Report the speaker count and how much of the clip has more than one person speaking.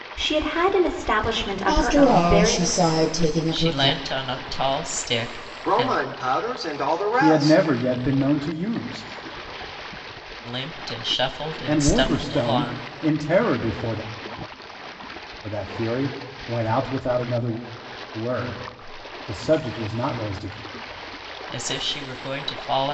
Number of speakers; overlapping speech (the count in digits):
5, about 16%